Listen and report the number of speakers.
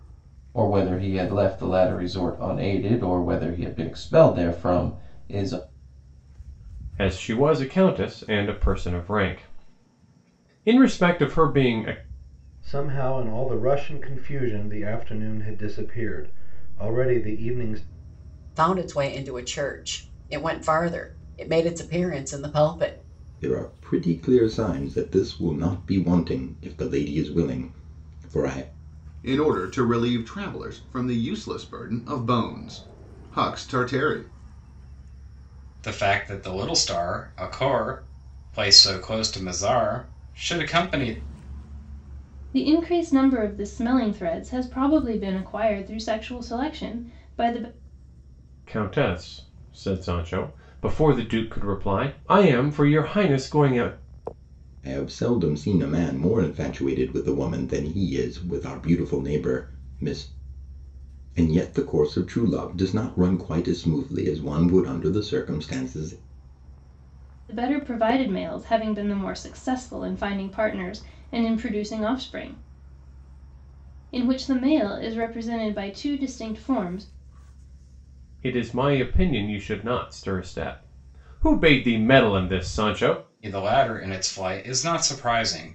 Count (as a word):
eight